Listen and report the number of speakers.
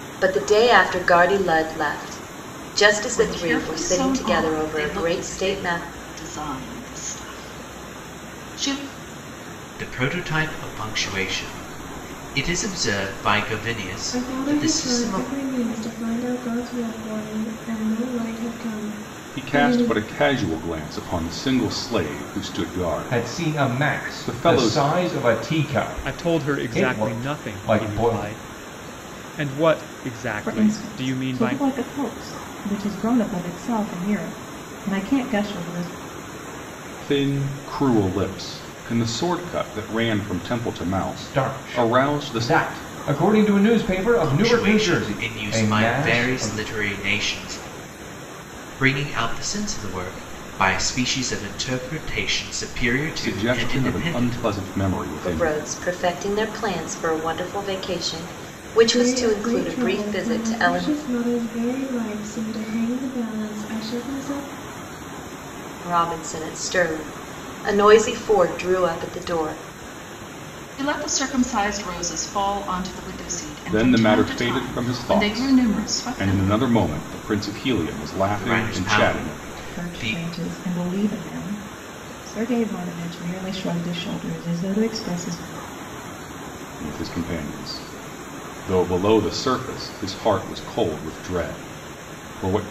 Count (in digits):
8